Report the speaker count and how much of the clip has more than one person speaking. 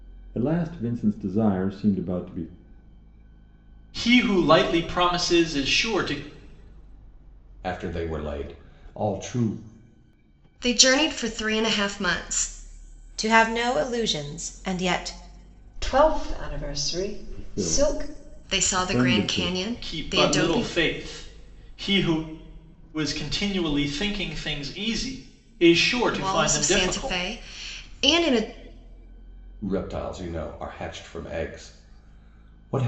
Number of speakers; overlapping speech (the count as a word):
six, about 12%